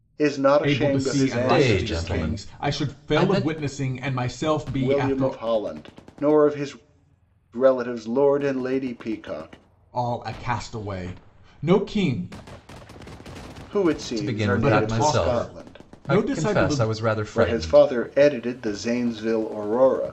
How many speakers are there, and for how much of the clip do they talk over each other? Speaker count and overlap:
3, about 34%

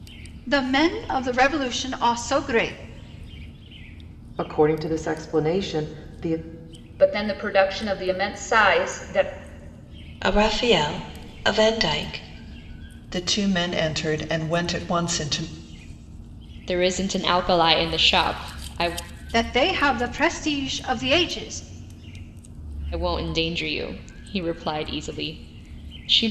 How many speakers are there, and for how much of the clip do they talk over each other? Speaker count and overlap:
6, no overlap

